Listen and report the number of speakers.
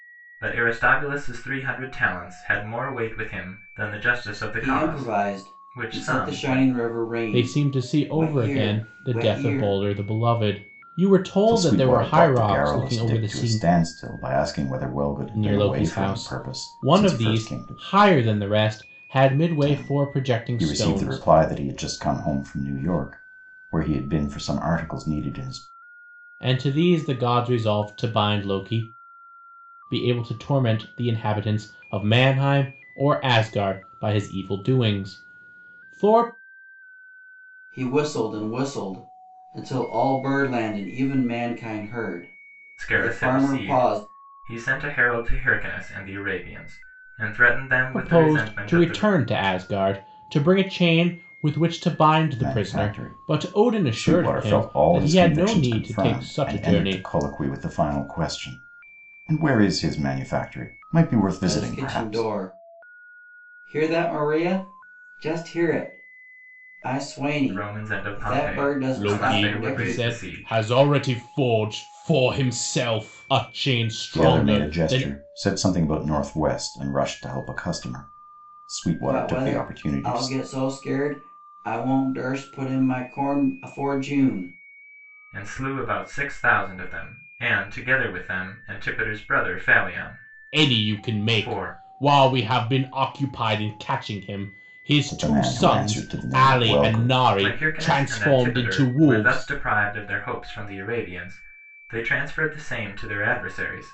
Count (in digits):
4